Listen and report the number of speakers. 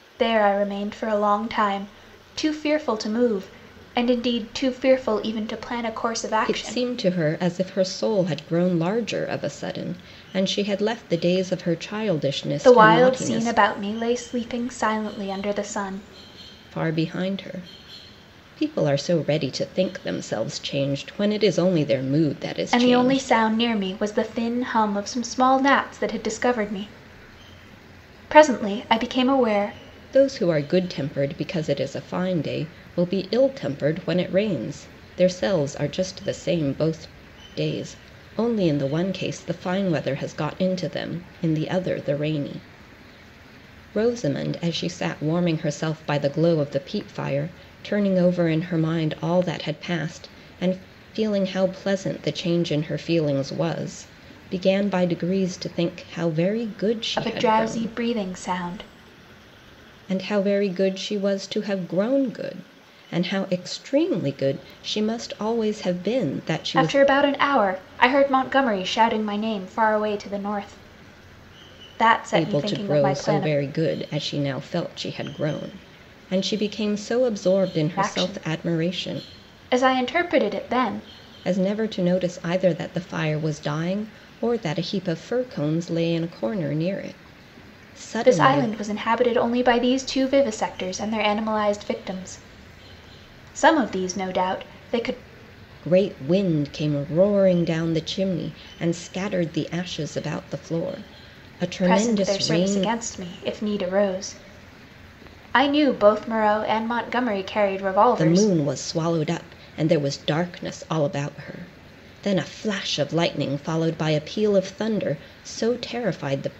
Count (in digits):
2